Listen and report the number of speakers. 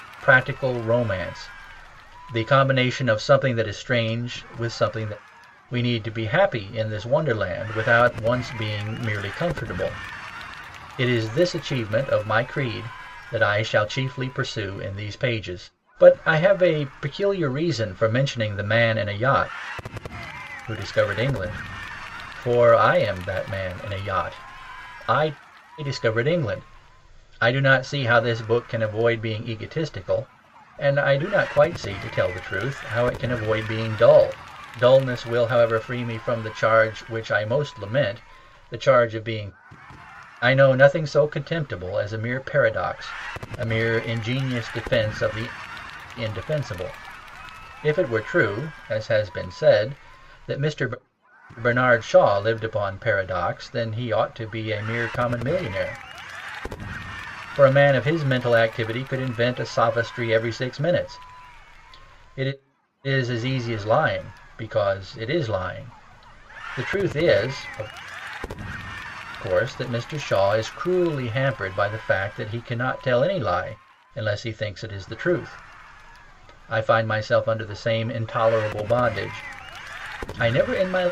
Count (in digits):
1